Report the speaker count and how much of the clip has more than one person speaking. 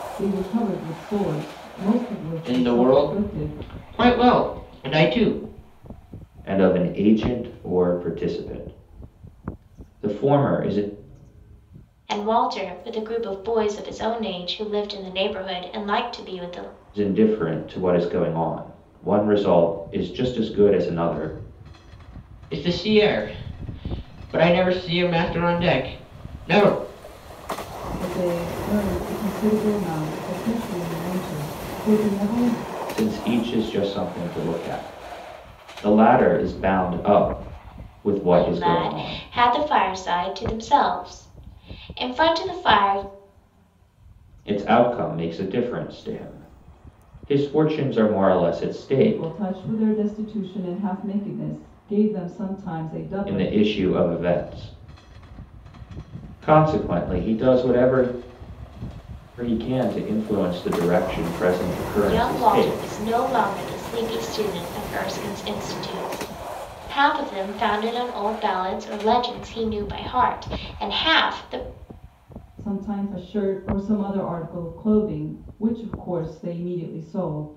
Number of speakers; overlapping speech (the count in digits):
4, about 5%